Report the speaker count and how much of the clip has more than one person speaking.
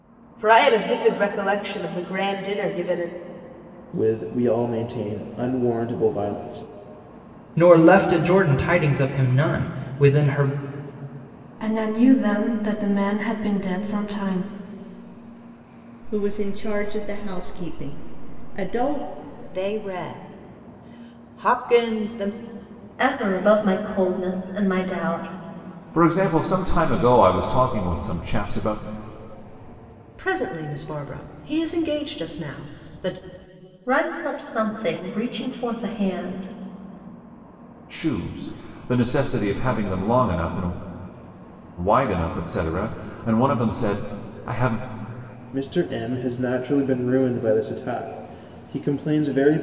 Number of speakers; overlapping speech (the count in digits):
9, no overlap